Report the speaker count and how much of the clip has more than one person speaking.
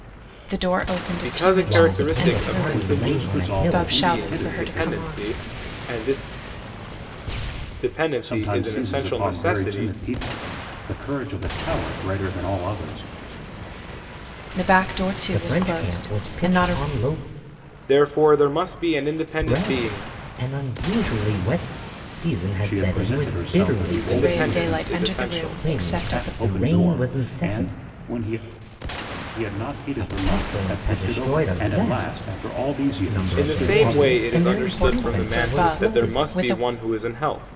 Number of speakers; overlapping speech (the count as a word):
four, about 51%